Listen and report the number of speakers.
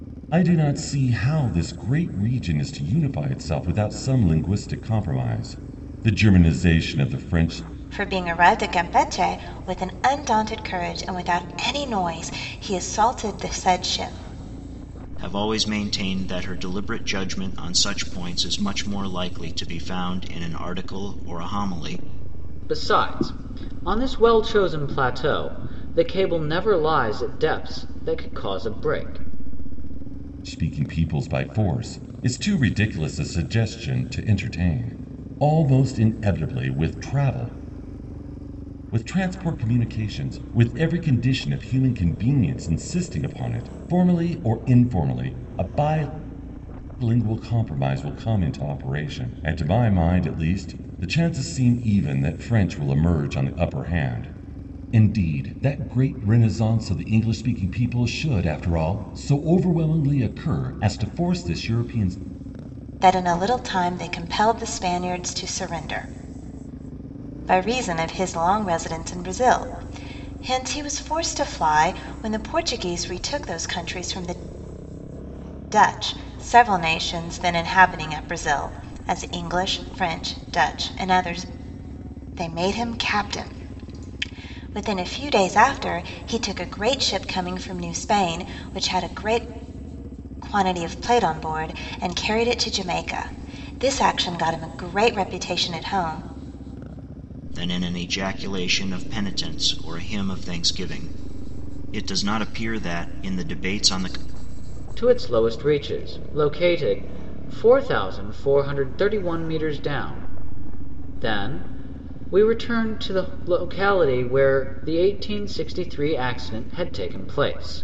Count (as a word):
four